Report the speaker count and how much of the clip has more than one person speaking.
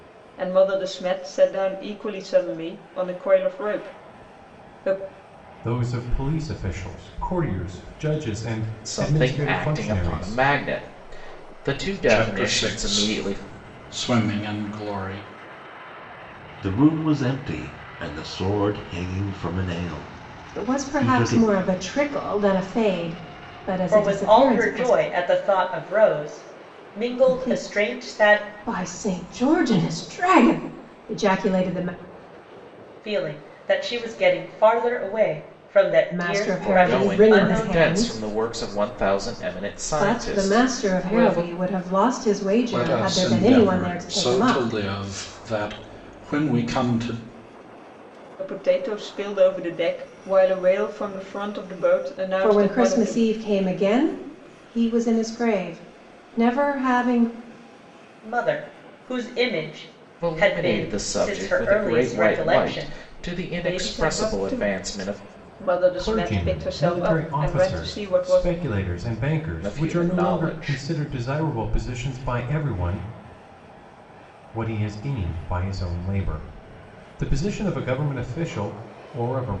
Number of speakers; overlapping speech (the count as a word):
seven, about 27%